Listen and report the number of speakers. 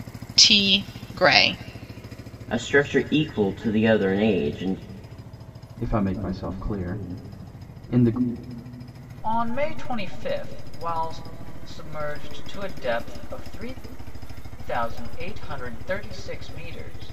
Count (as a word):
four